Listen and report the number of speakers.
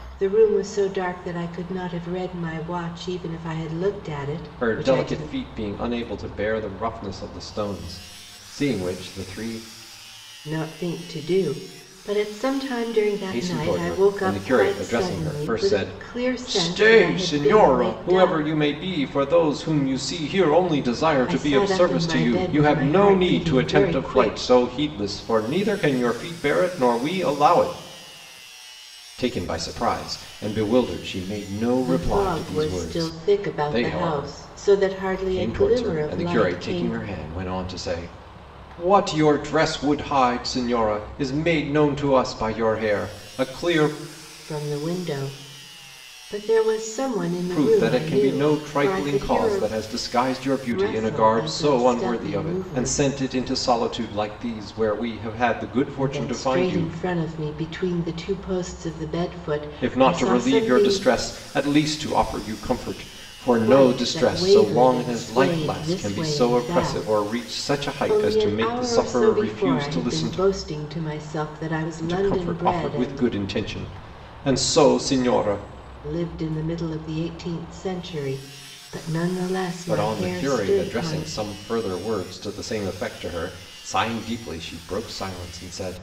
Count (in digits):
2